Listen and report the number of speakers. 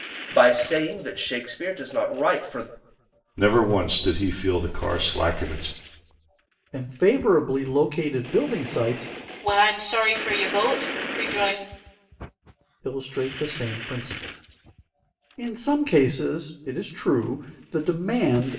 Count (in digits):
4